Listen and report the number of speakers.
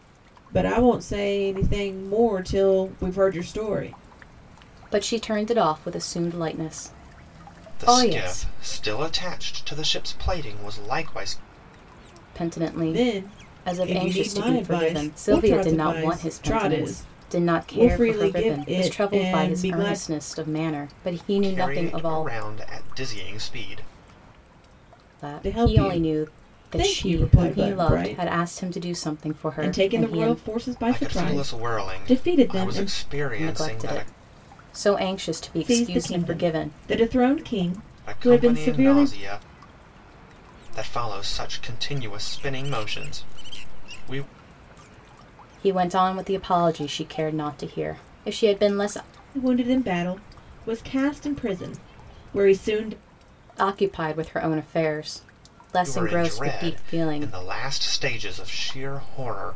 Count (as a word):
three